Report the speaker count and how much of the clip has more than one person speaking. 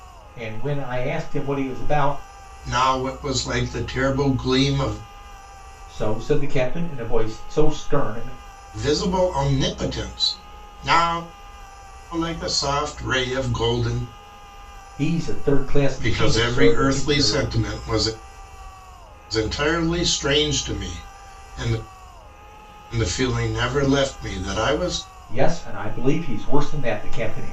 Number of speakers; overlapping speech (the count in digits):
2, about 5%